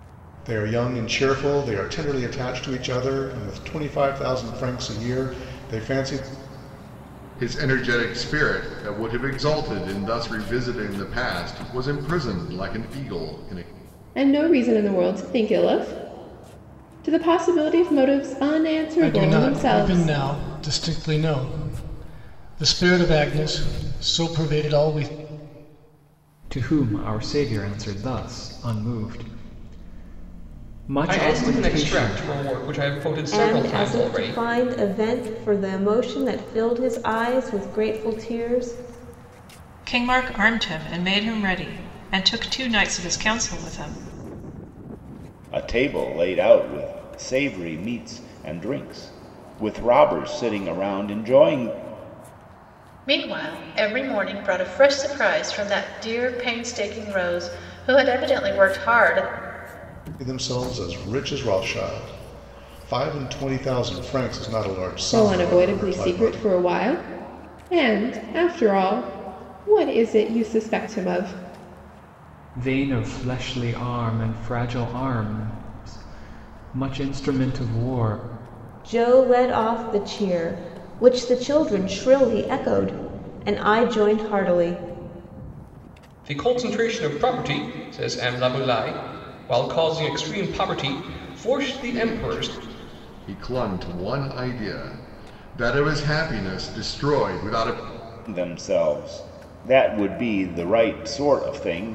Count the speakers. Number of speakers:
ten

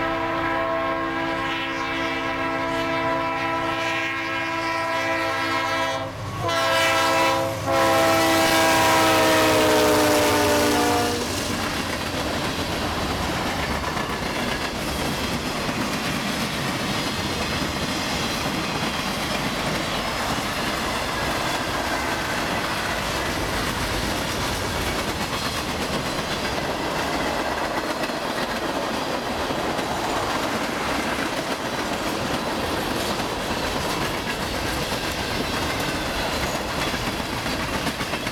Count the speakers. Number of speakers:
zero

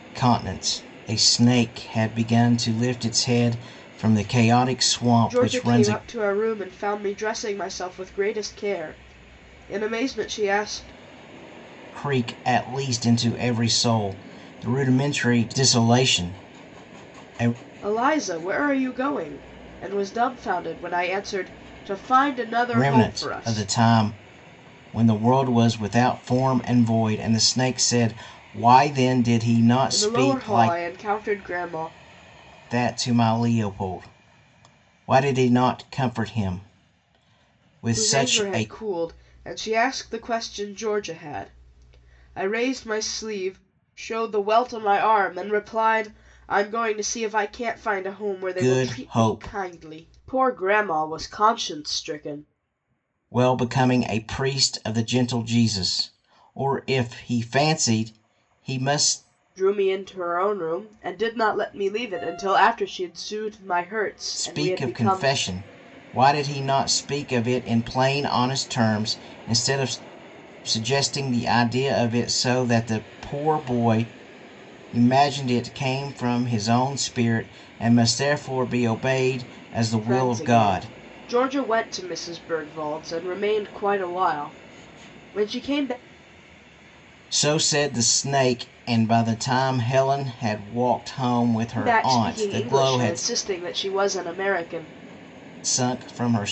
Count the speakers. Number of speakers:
two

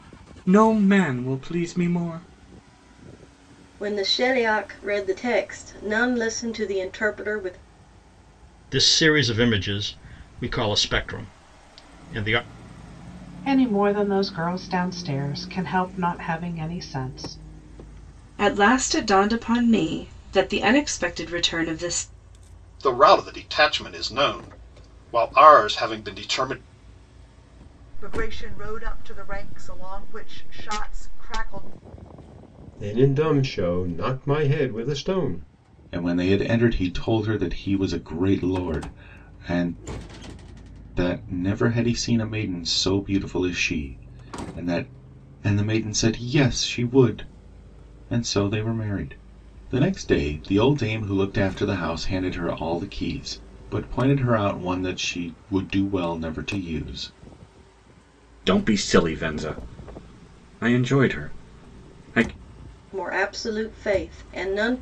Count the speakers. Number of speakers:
nine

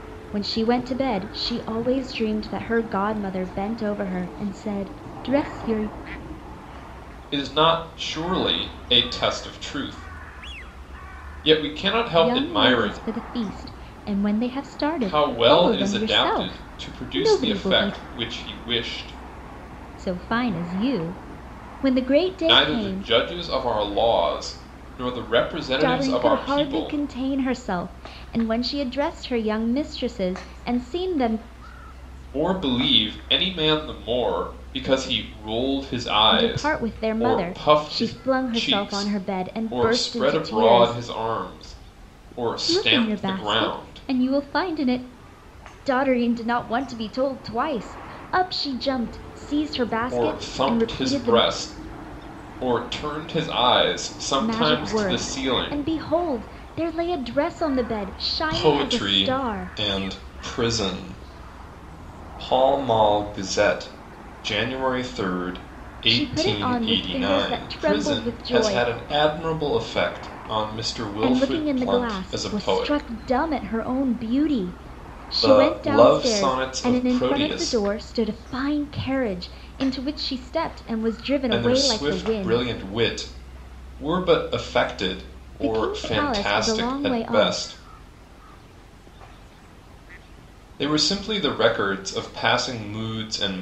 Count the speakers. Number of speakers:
two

